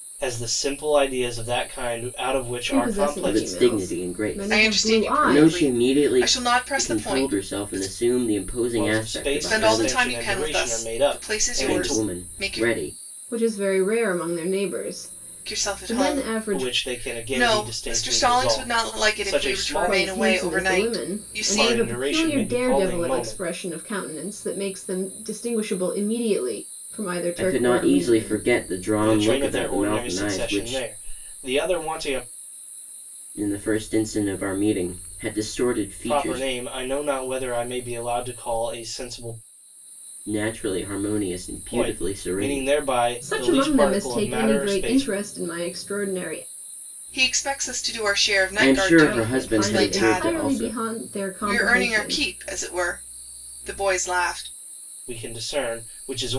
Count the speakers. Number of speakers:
four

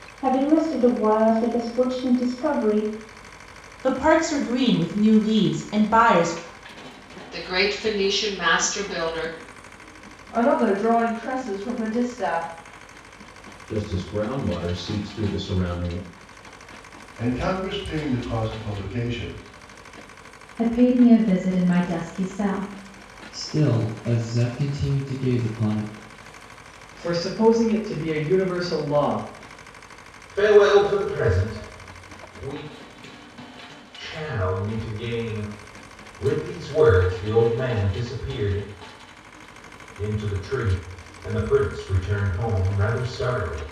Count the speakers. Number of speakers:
ten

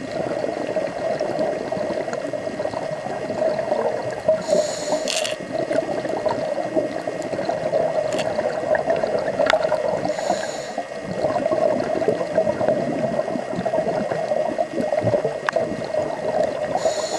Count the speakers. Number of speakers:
zero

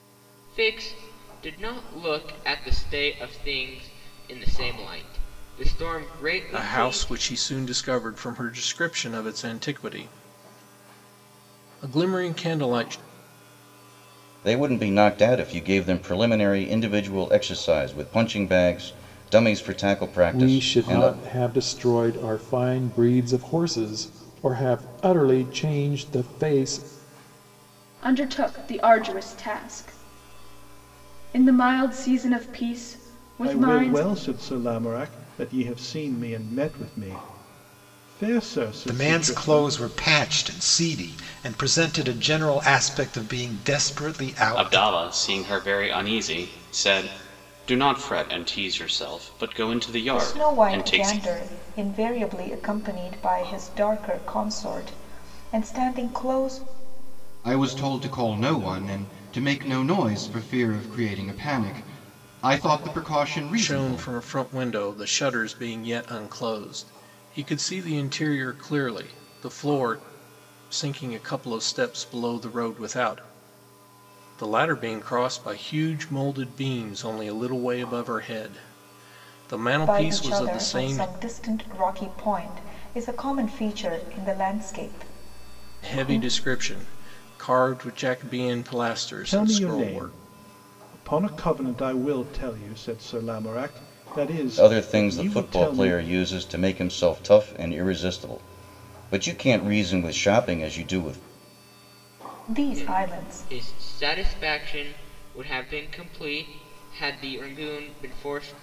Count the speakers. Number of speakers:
ten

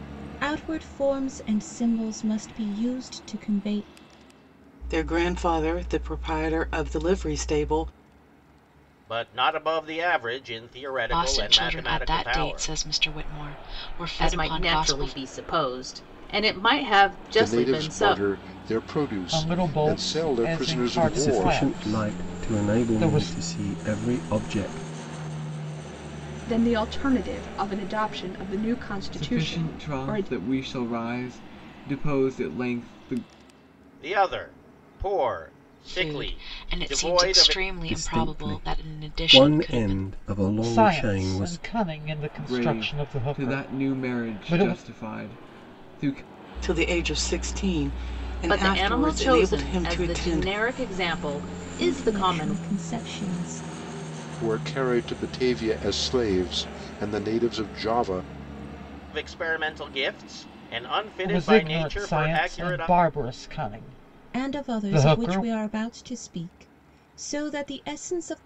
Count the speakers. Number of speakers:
ten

